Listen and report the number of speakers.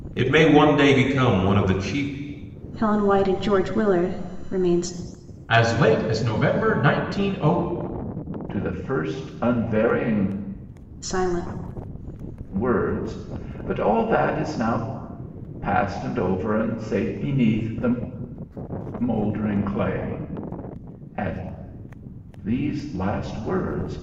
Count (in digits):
4